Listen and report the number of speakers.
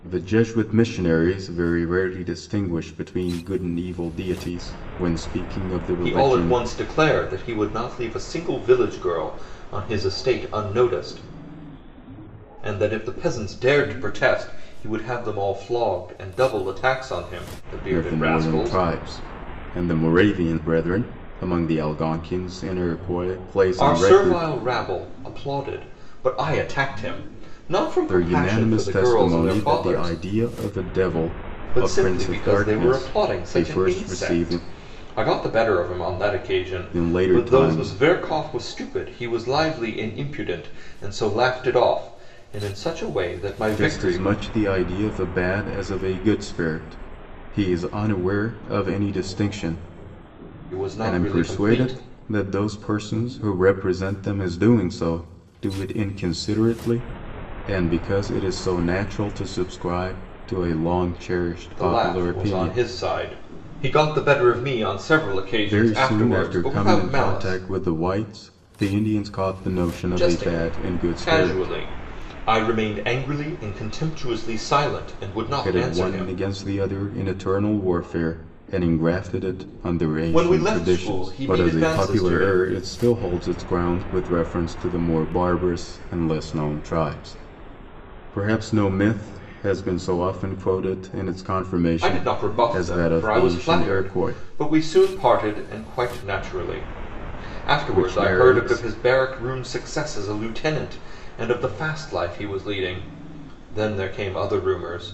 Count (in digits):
2